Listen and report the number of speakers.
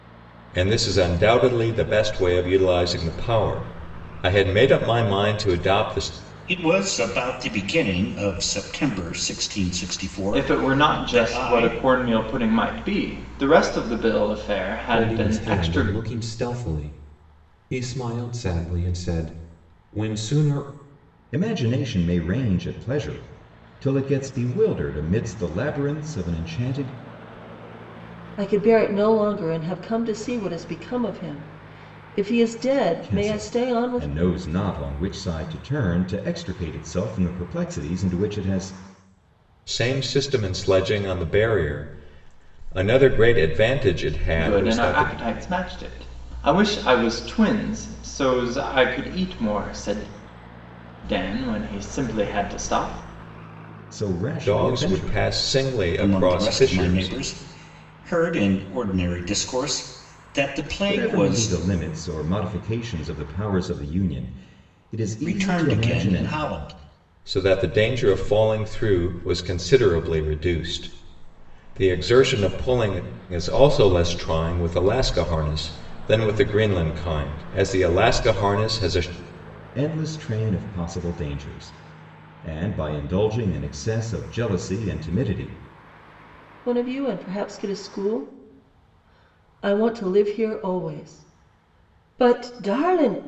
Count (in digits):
6